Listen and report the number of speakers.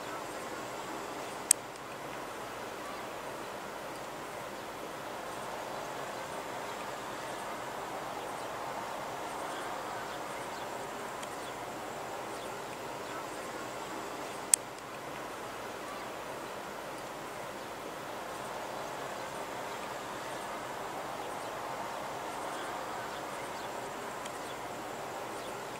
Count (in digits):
0